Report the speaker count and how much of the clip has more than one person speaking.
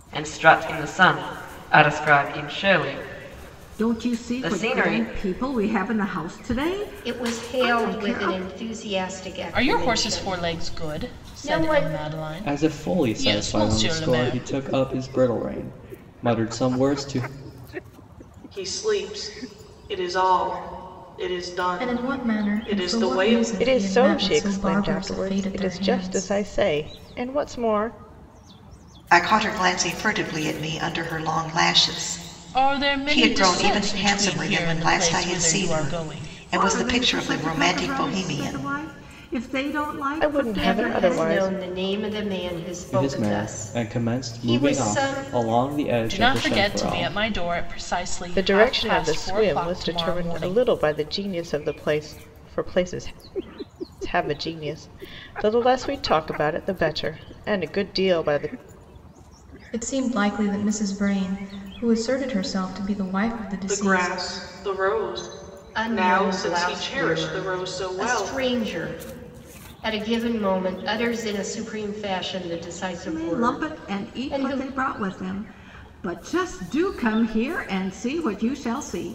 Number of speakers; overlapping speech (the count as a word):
nine, about 38%